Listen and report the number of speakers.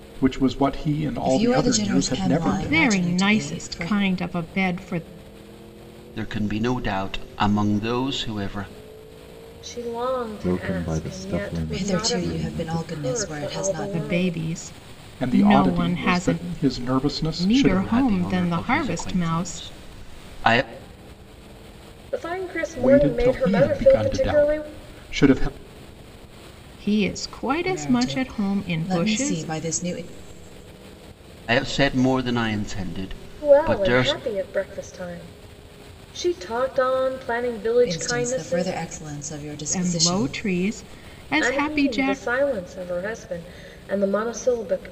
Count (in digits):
6